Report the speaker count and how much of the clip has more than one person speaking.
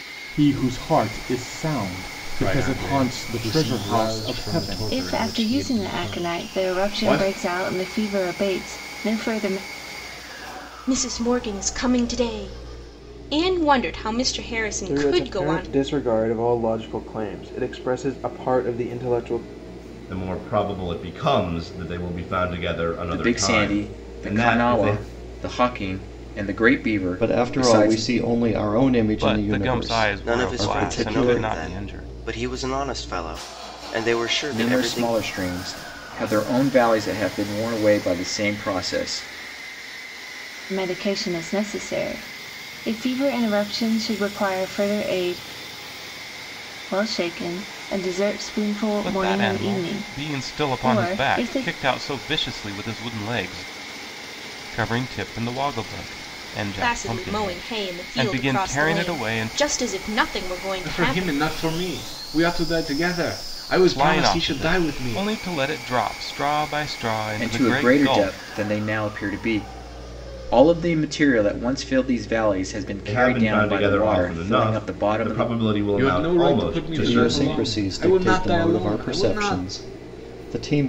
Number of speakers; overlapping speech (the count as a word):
ten, about 34%